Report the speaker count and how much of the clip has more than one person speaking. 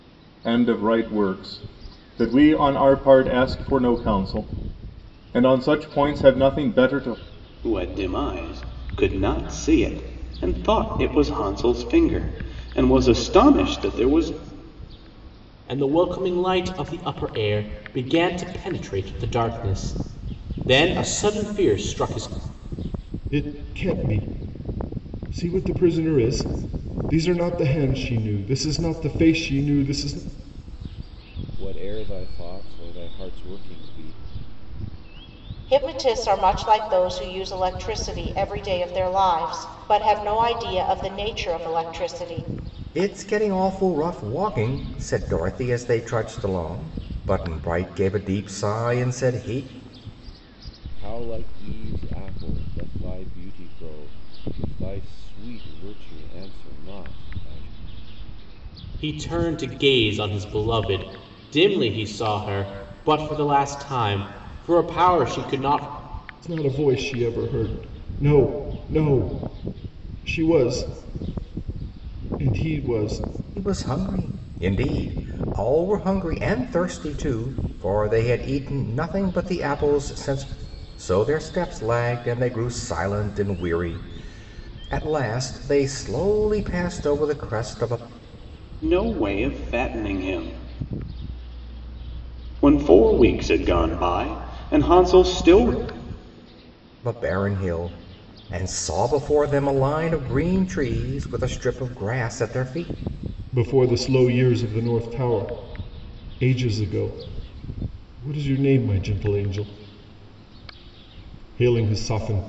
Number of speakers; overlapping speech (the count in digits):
7, no overlap